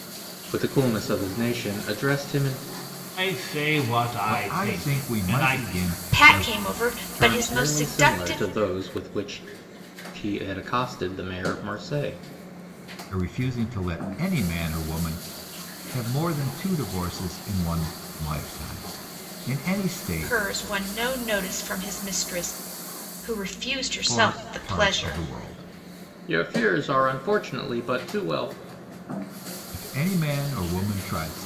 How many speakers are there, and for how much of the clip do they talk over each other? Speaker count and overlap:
4, about 15%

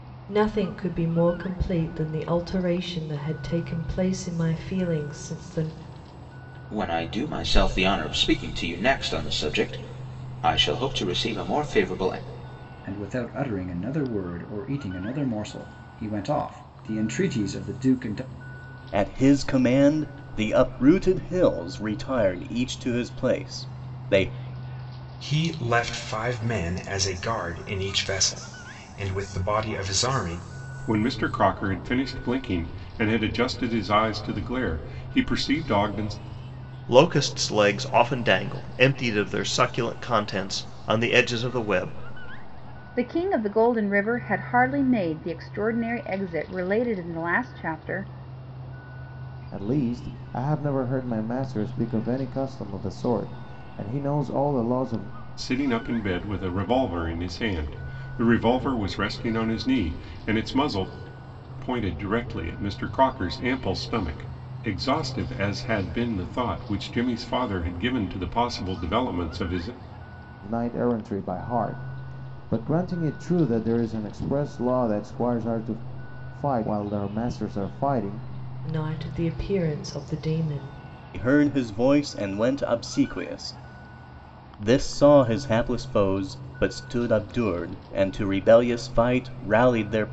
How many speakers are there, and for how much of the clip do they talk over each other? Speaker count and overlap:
9, no overlap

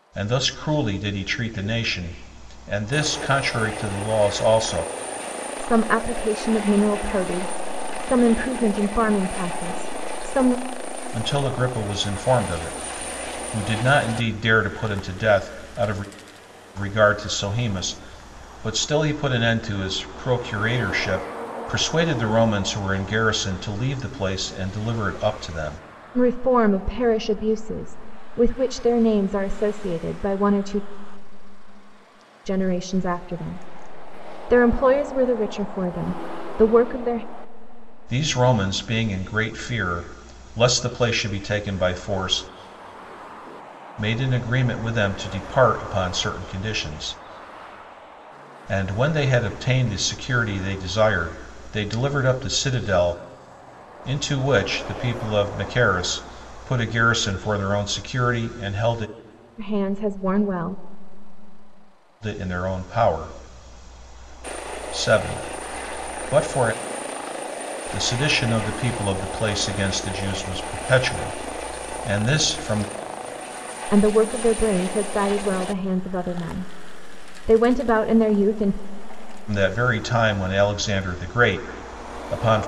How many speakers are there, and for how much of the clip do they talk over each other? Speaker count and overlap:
2, no overlap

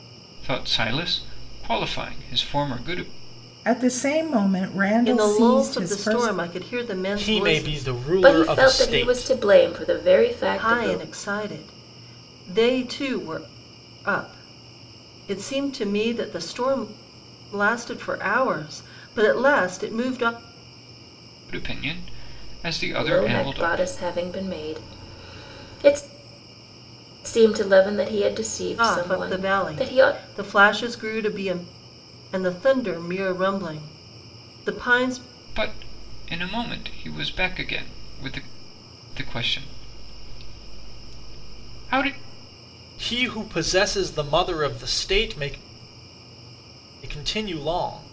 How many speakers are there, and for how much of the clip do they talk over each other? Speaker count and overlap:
5, about 13%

